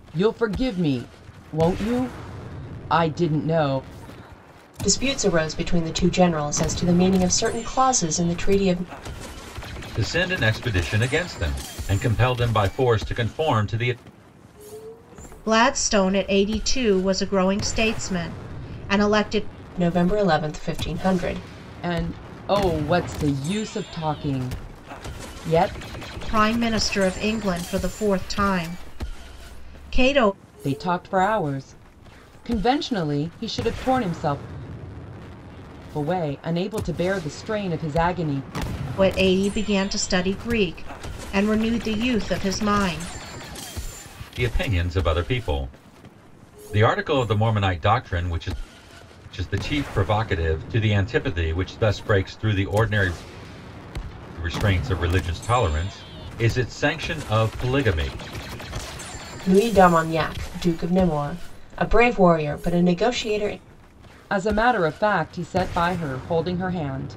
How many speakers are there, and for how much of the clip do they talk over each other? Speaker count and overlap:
4, no overlap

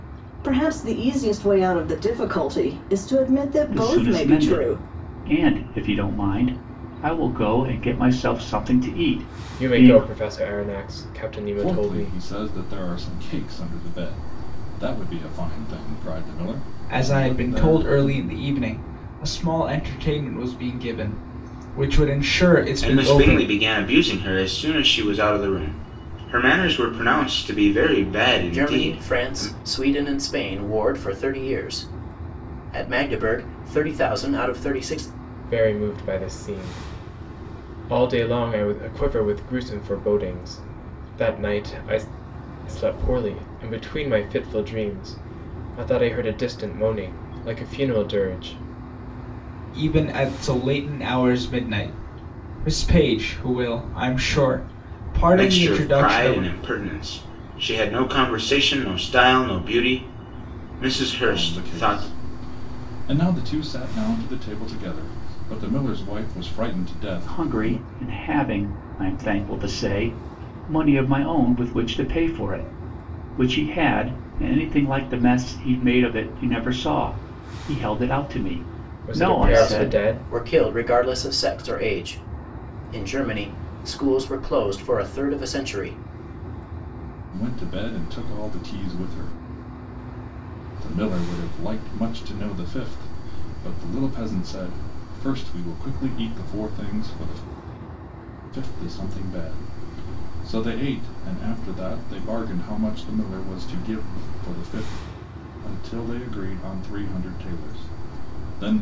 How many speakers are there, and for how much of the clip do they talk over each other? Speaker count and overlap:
7, about 9%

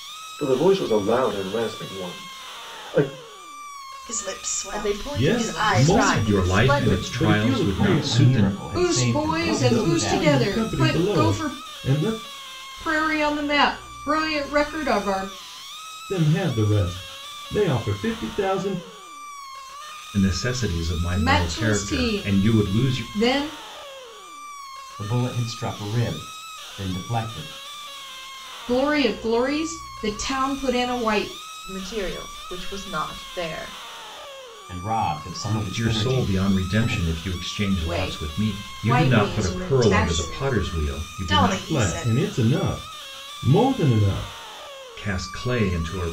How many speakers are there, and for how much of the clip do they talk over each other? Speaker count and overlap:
7, about 31%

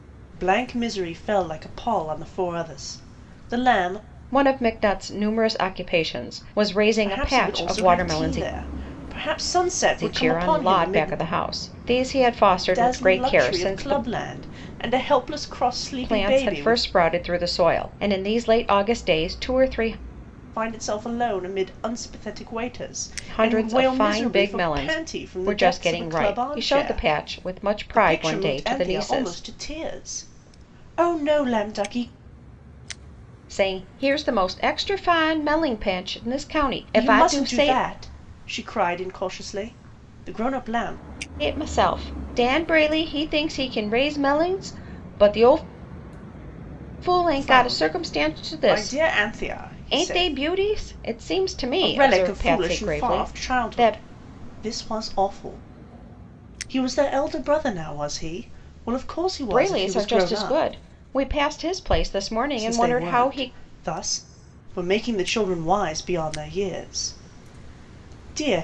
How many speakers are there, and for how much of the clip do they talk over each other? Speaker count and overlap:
2, about 25%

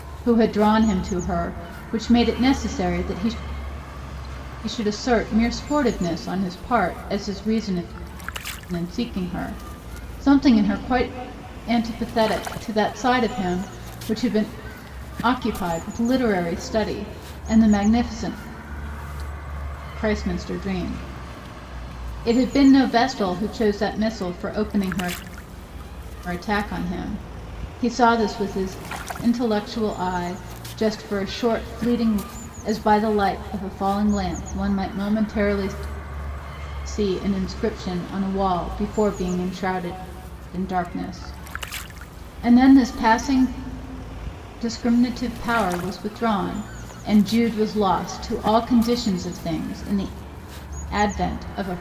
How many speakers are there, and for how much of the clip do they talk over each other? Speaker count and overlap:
1, no overlap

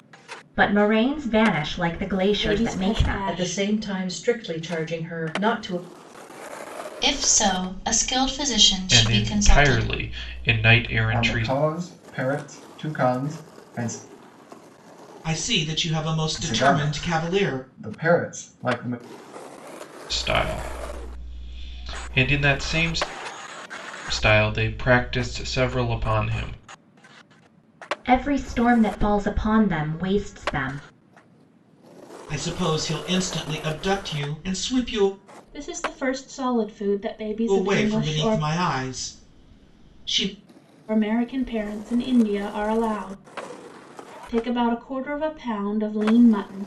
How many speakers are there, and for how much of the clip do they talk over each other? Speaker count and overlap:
7, about 10%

